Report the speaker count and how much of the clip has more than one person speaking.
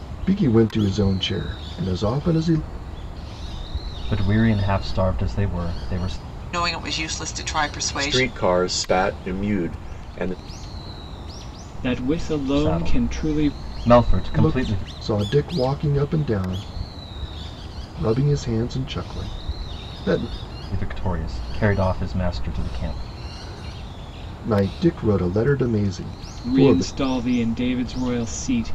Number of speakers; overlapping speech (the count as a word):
five, about 8%